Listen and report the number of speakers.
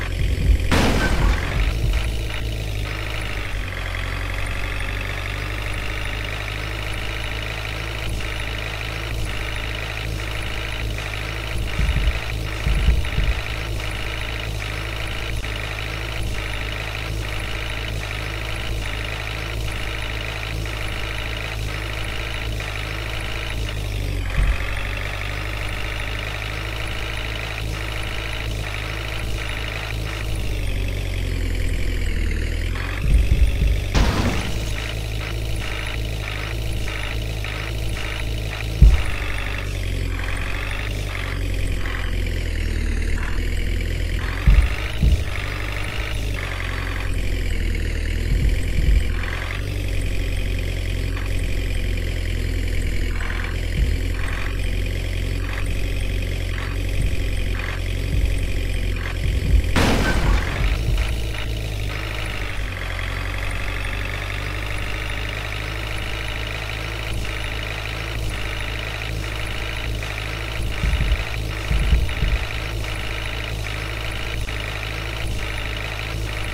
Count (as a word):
zero